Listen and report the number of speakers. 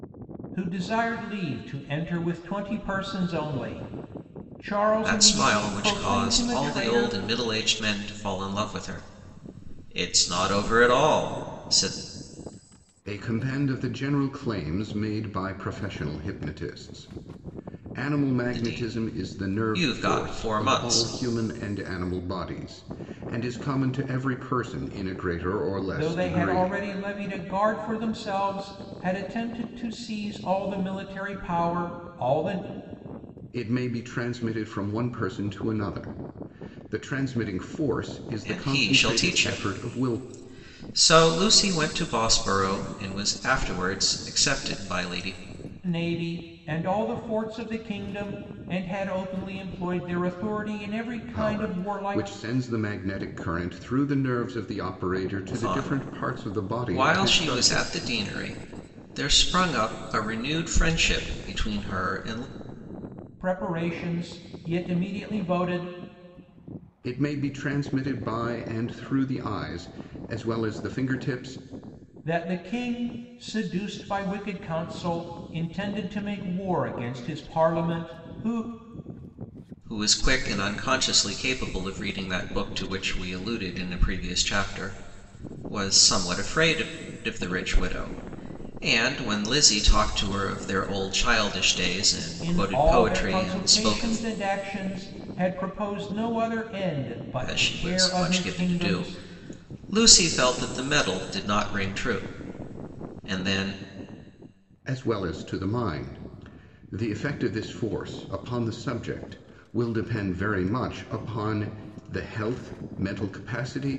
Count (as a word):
three